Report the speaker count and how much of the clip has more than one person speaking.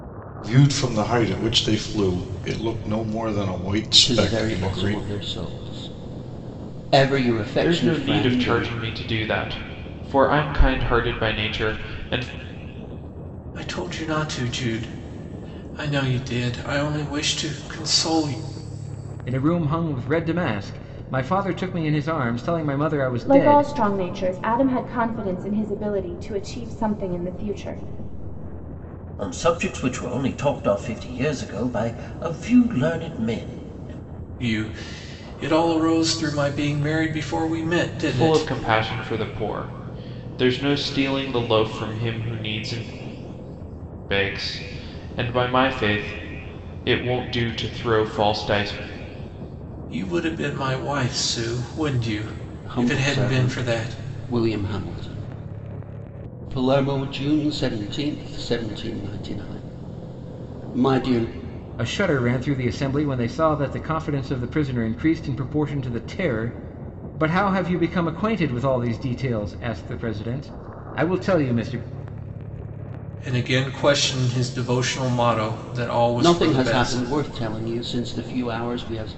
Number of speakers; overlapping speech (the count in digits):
7, about 7%